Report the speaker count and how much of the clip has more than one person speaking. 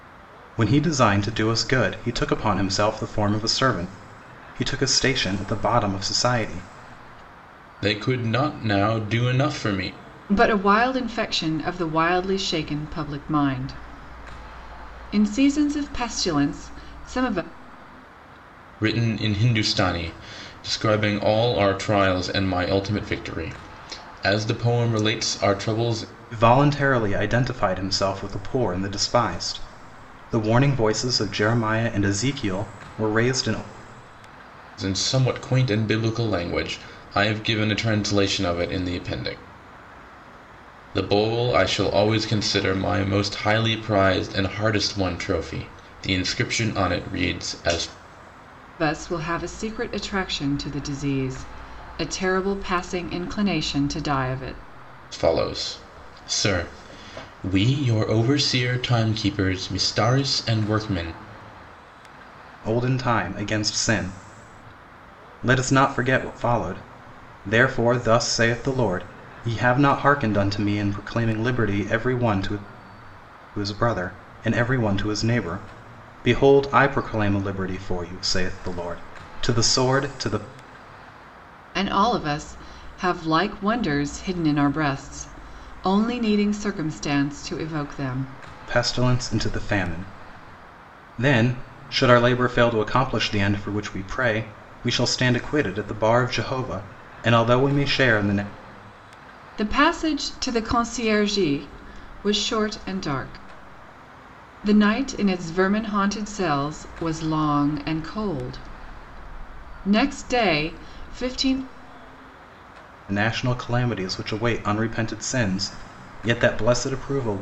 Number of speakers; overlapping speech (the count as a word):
three, no overlap